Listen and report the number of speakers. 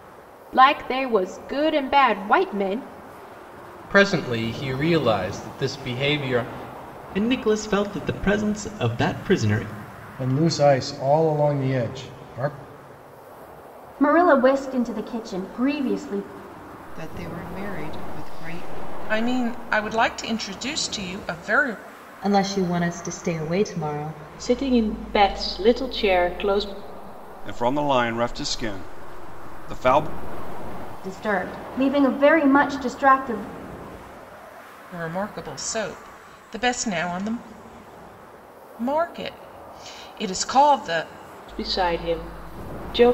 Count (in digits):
10